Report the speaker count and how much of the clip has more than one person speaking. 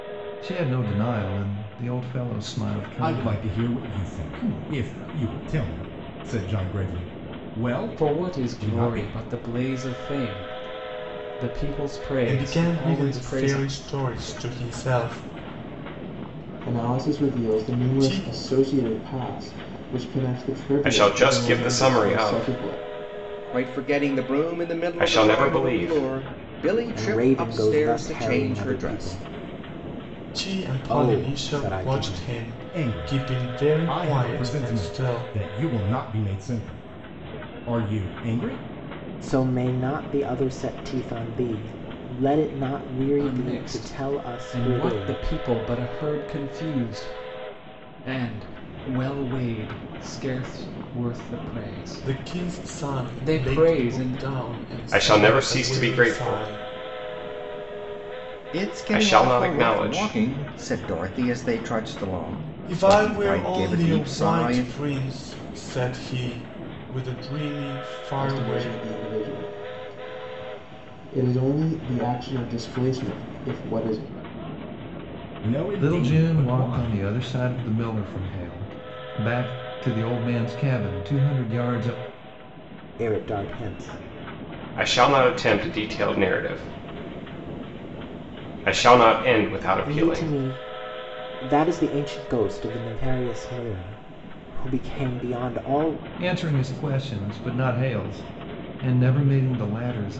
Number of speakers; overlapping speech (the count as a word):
eight, about 30%